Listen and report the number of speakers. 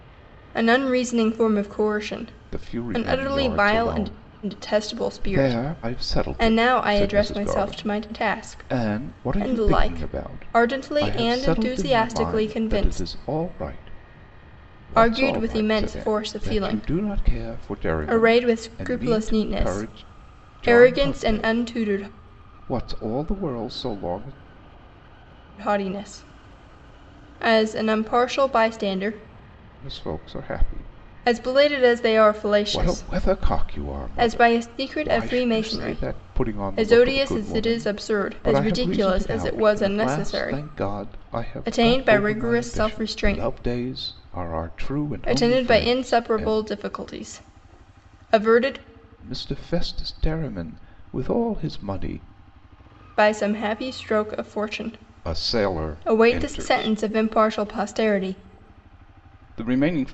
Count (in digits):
2